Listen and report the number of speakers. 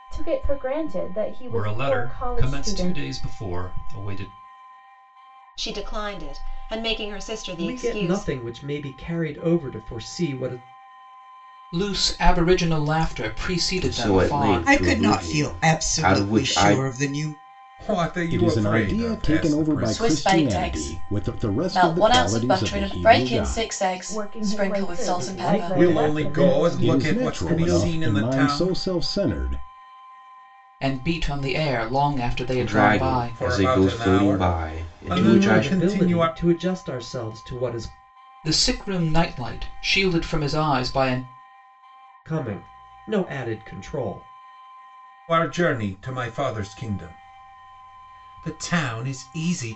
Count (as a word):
ten